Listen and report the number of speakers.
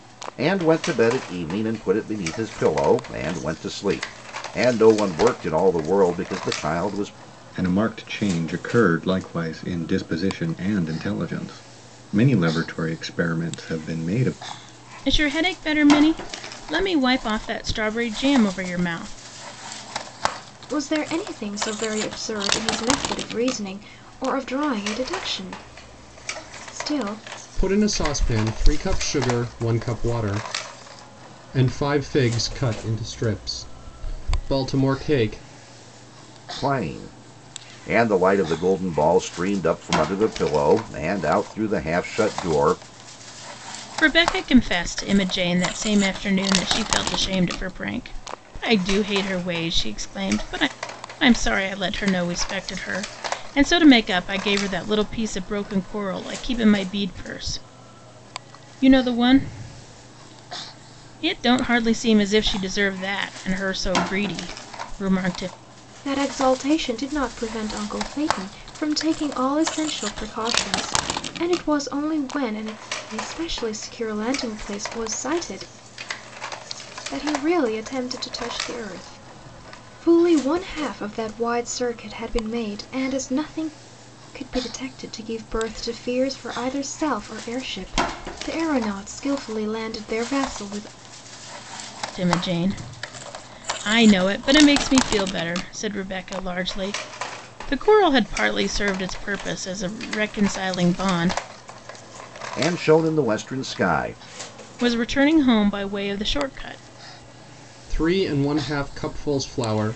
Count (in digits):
5